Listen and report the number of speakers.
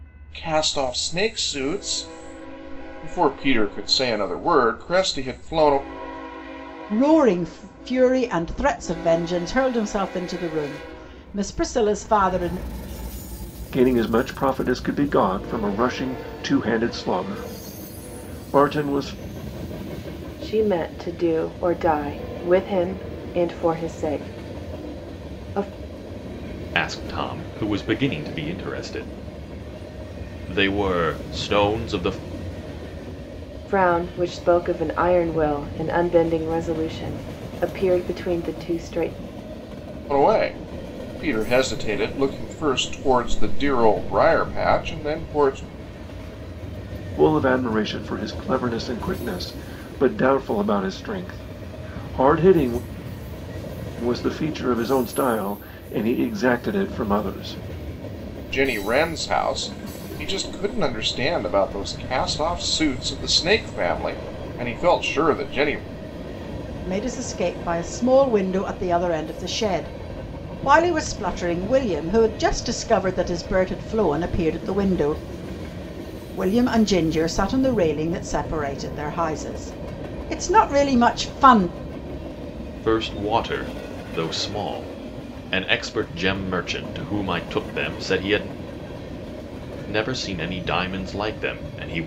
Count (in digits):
5